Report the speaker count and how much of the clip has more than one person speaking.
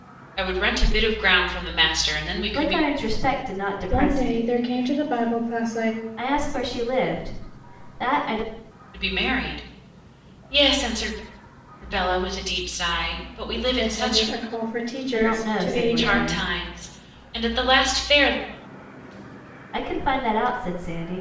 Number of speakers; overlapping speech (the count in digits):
3, about 13%